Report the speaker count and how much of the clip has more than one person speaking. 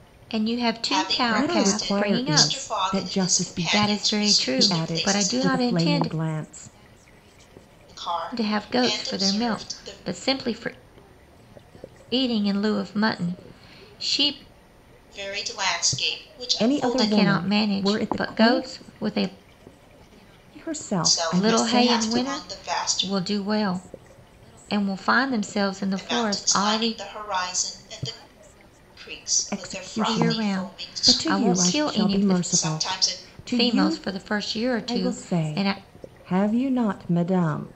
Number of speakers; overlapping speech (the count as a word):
three, about 46%